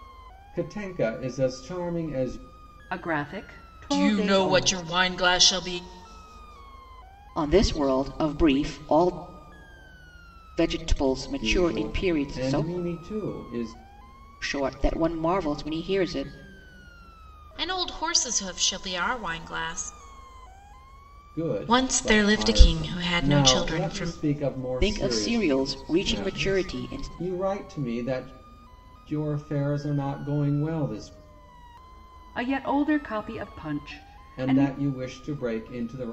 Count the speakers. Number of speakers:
four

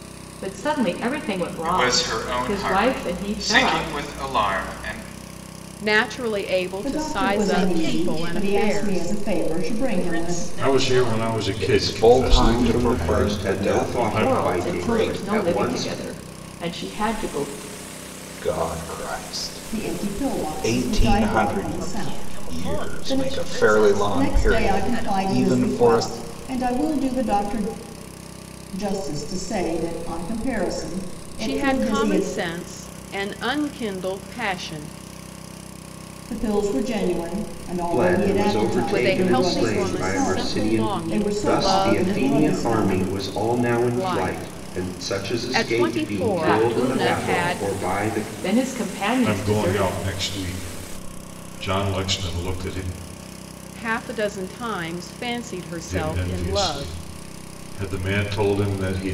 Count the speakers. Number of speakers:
eight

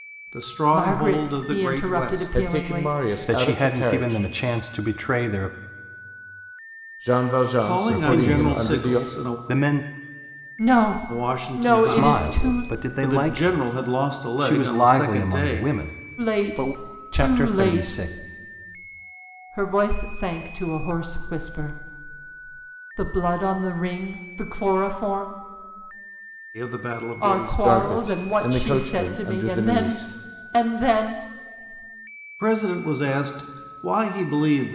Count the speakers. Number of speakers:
four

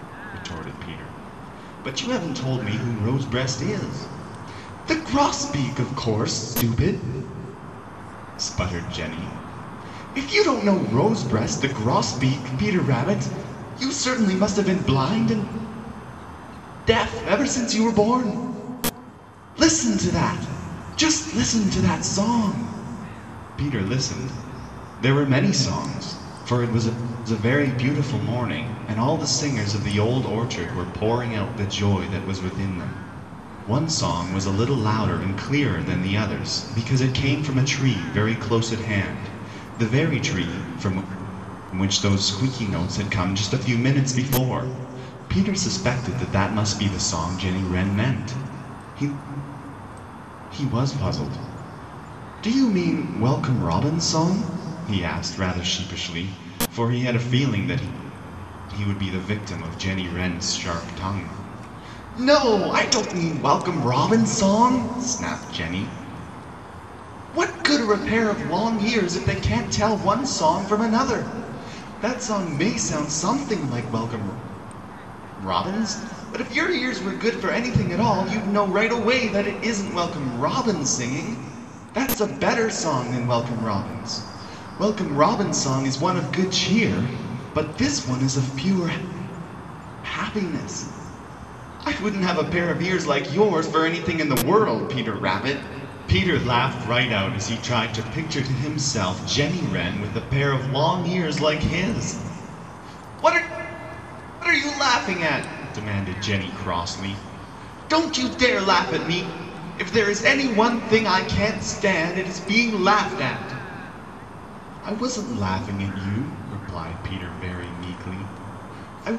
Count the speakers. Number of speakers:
one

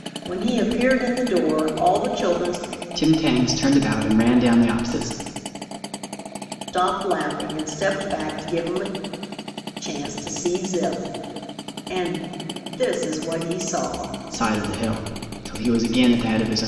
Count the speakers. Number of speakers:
two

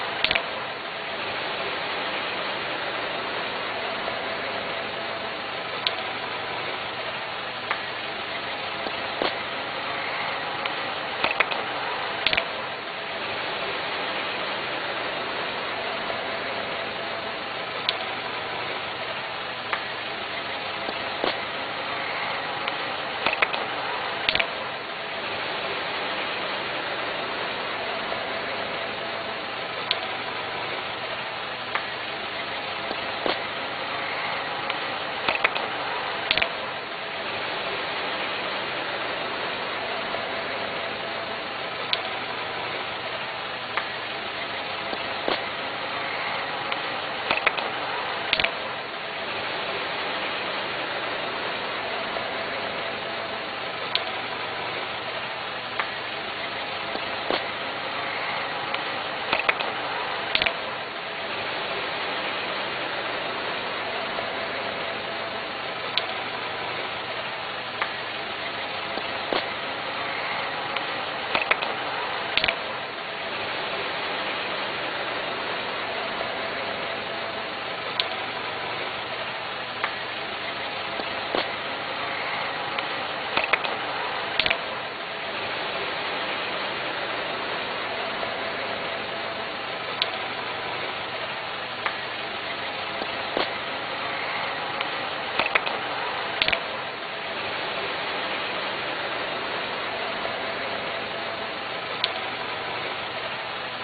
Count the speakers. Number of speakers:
zero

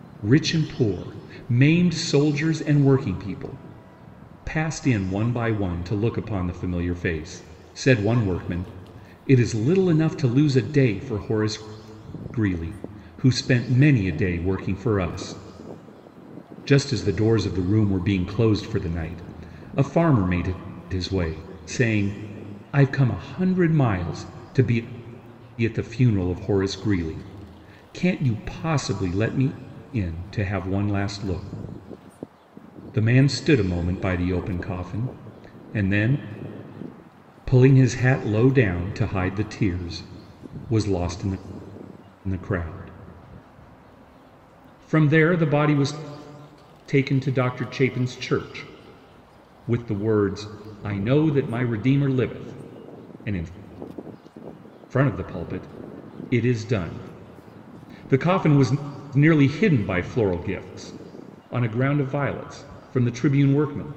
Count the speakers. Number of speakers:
one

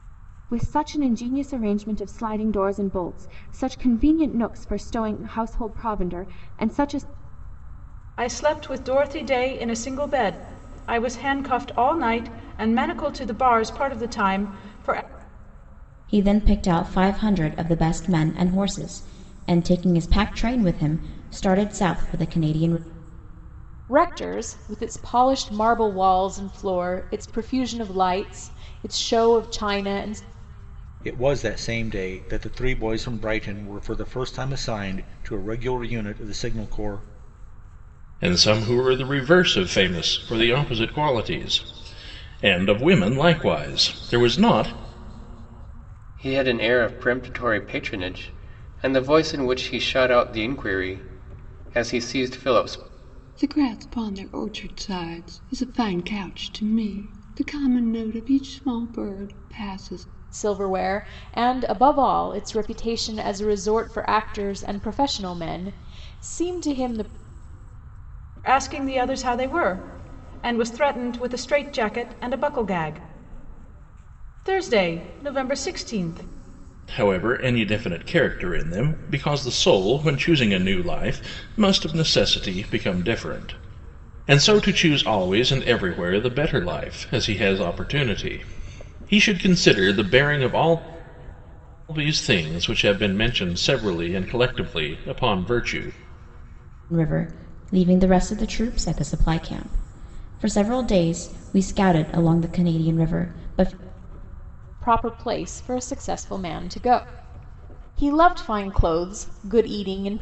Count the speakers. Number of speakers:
eight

